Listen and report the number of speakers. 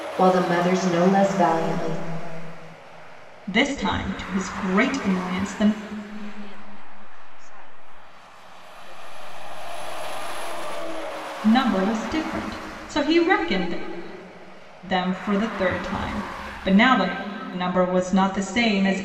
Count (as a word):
three